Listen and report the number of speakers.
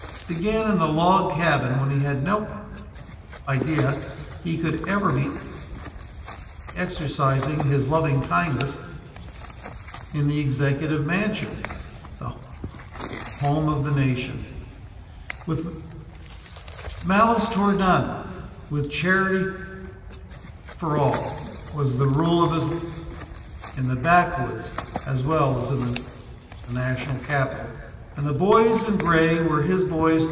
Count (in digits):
1